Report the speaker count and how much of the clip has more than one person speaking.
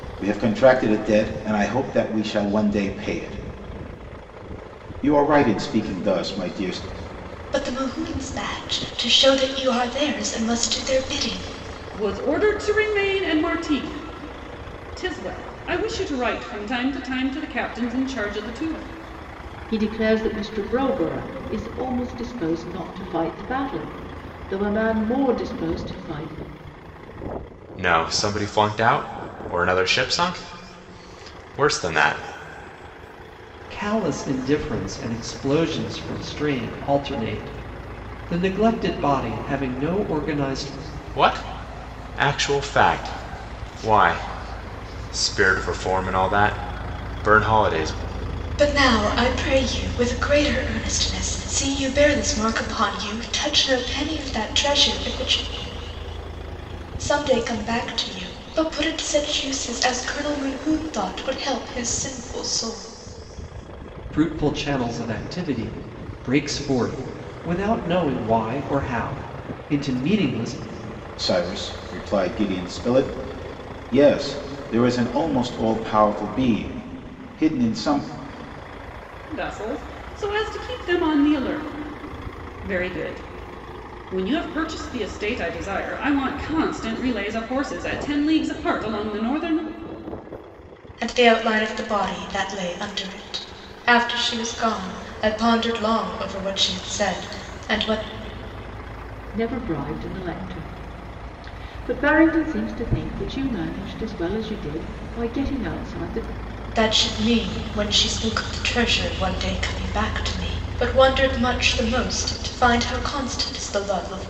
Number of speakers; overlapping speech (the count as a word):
six, no overlap